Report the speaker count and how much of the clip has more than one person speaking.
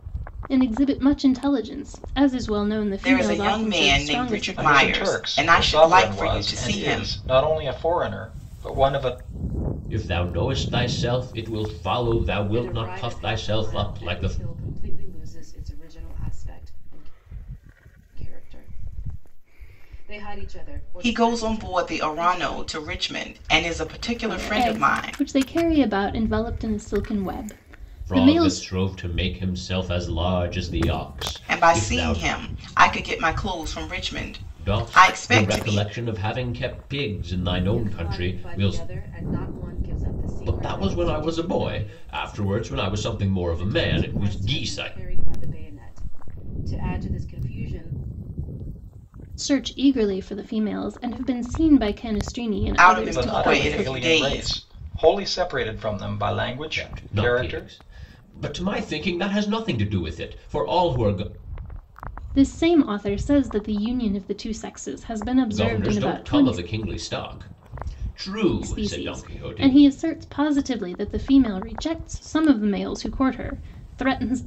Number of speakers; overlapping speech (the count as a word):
five, about 28%